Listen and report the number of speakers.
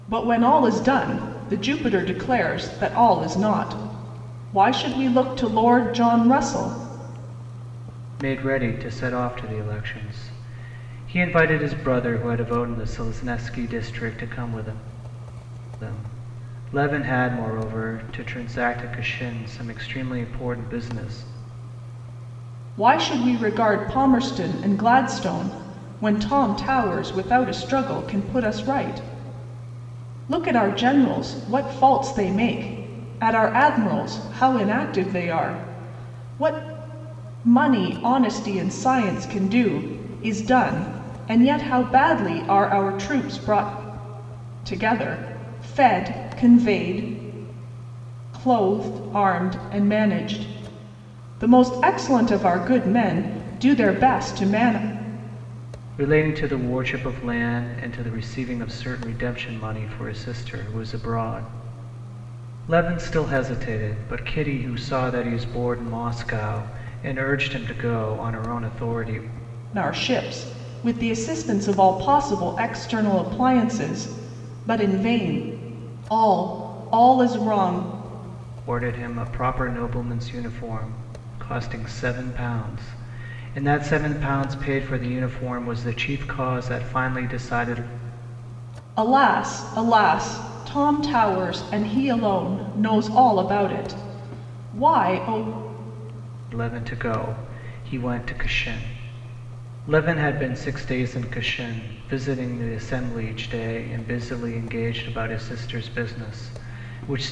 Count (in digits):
2